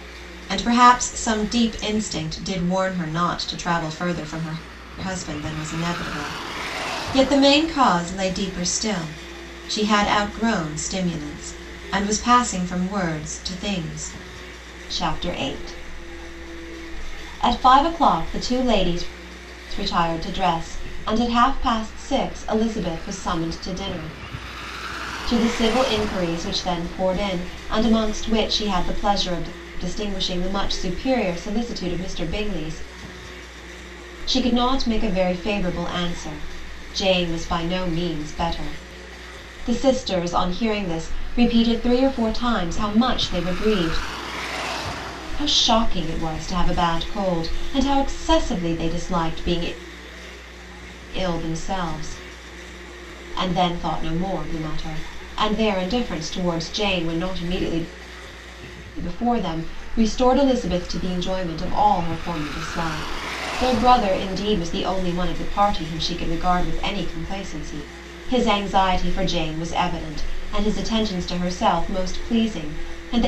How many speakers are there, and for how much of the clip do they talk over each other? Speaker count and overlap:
one, no overlap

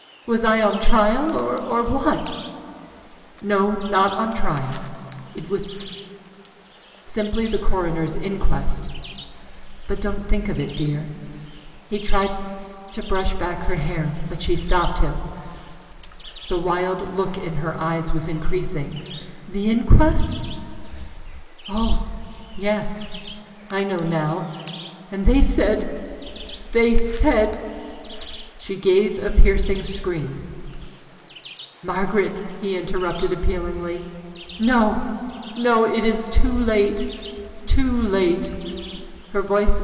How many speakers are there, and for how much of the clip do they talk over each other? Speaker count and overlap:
one, no overlap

